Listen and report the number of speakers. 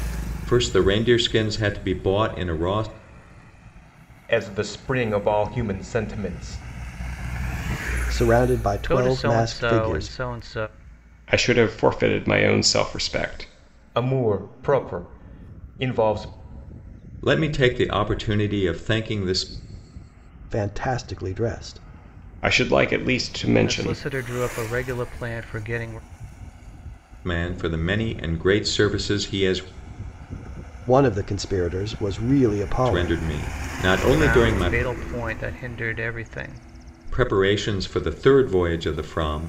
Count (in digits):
5